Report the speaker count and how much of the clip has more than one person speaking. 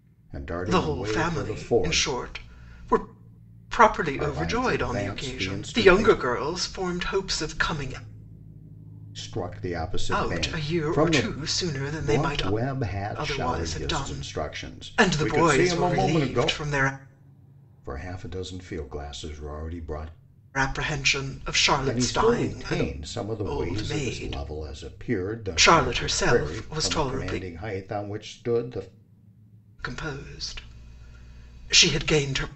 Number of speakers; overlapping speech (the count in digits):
2, about 37%